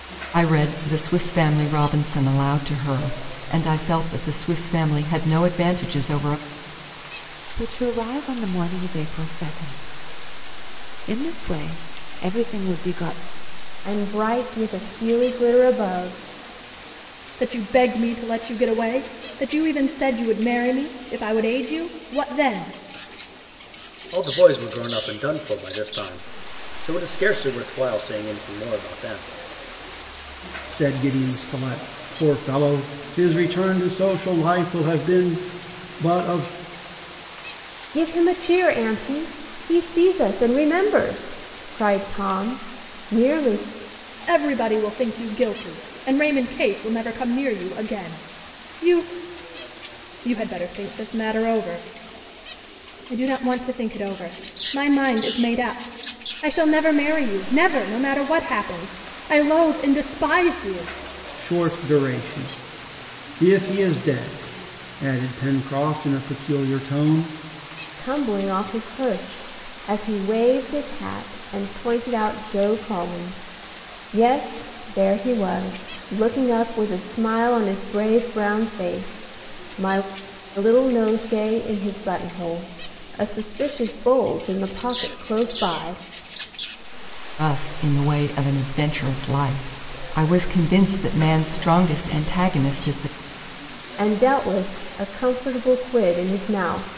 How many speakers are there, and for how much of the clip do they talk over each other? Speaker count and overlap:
six, no overlap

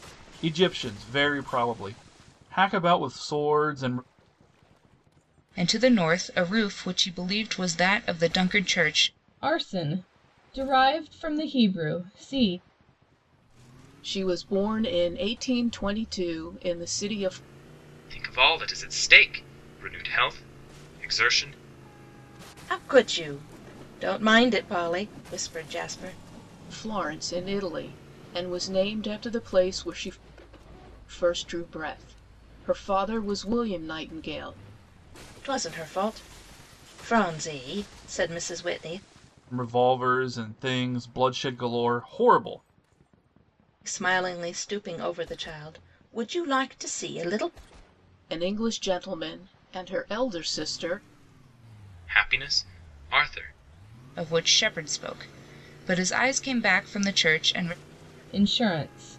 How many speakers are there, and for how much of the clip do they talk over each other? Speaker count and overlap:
six, no overlap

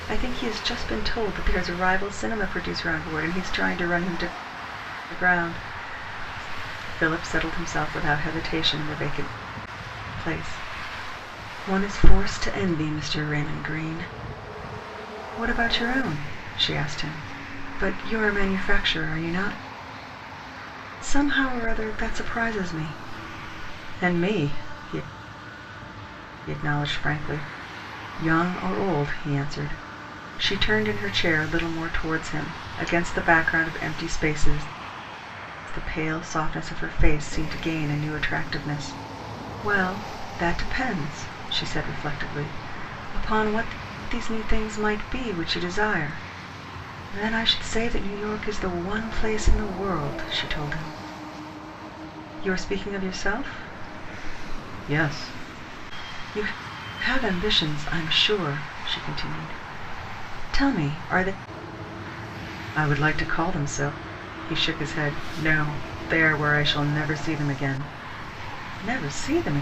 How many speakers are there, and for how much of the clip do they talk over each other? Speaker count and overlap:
one, no overlap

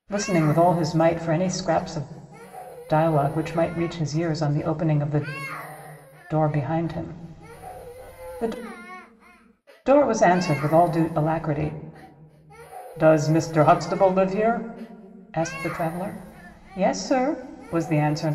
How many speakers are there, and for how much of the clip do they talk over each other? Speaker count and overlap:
one, no overlap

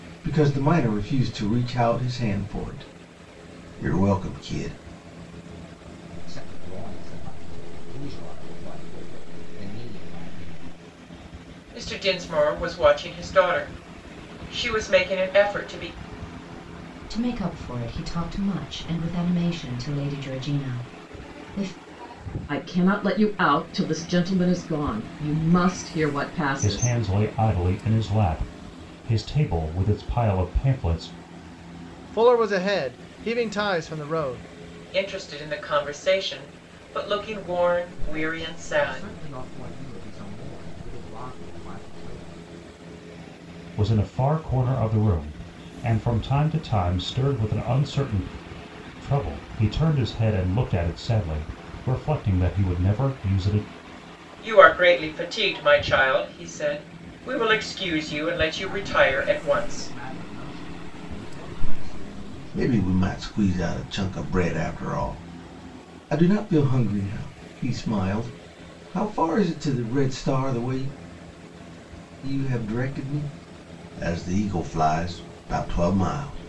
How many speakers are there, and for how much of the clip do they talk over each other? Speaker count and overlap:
seven, about 4%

